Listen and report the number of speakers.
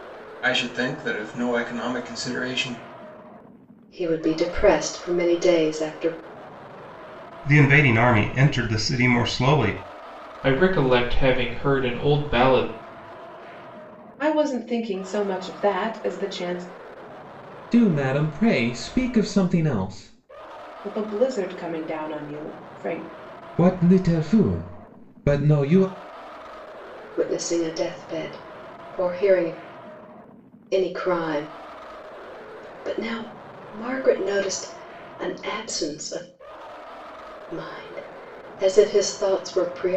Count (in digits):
6